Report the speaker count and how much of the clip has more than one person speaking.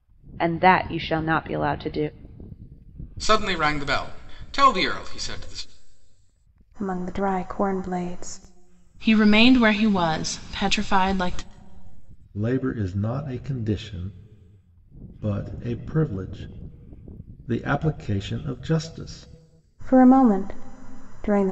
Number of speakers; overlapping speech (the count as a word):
five, no overlap